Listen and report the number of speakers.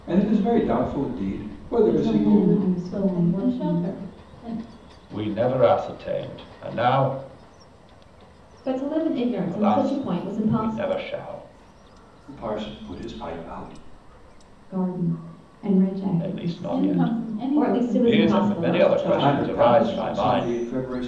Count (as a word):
five